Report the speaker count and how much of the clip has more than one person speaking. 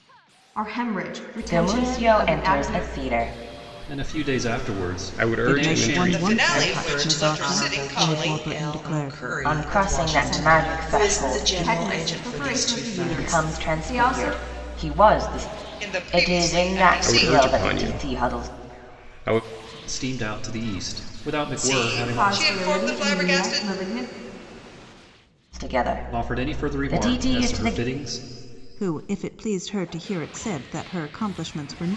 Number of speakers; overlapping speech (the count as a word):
seven, about 53%